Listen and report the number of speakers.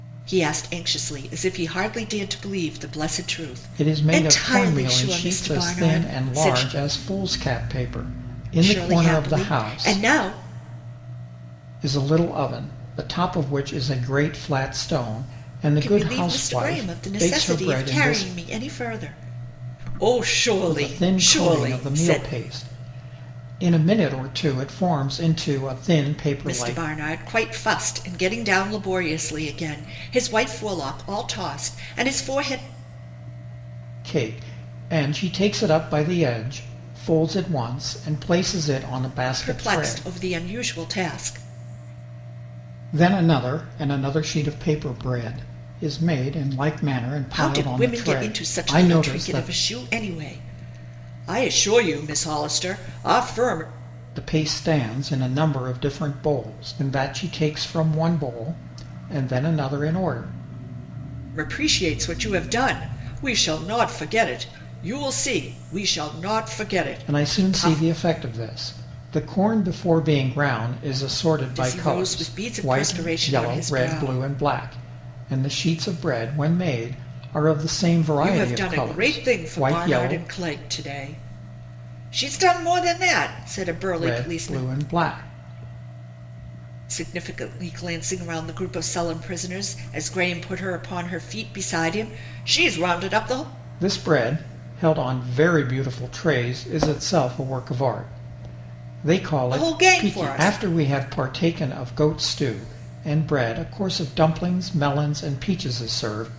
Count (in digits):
2